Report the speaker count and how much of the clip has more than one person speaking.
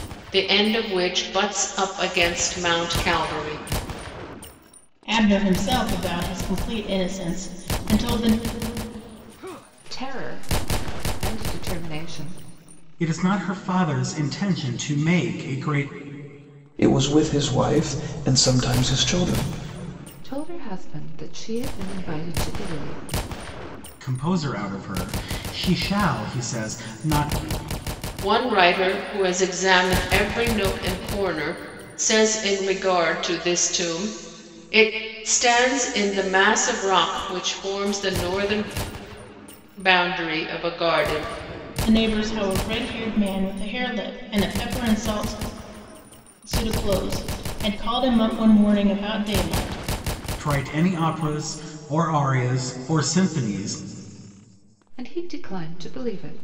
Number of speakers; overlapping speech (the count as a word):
five, no overlap